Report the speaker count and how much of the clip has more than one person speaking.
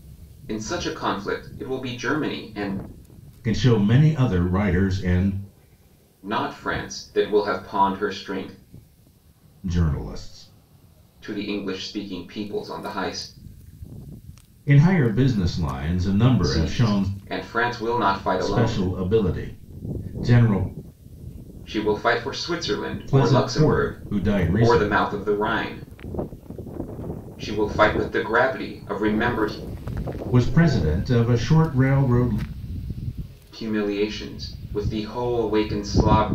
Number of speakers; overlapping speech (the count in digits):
2, about 7%